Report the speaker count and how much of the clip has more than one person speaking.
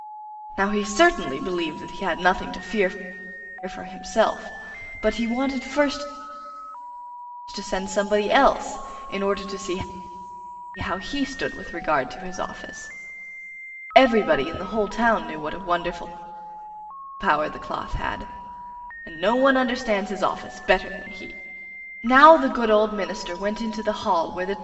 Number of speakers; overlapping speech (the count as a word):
one, no overlap